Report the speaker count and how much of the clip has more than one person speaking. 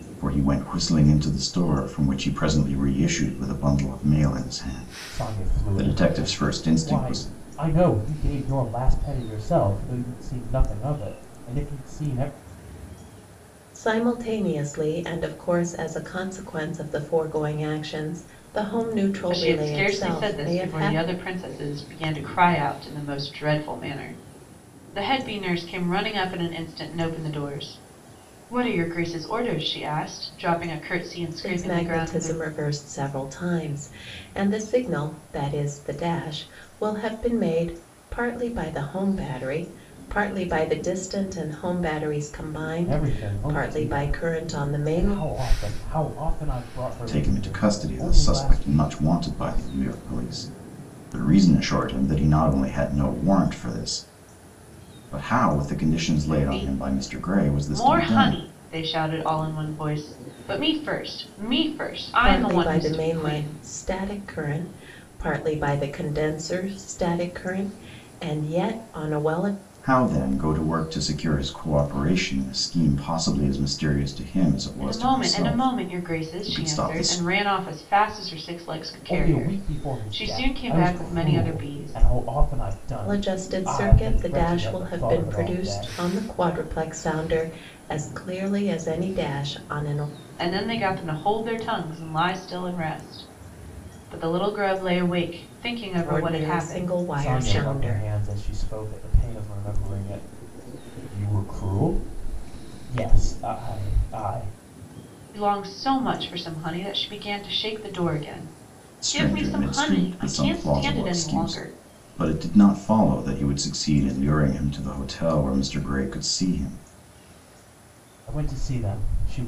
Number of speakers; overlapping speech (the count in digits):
4, about 22%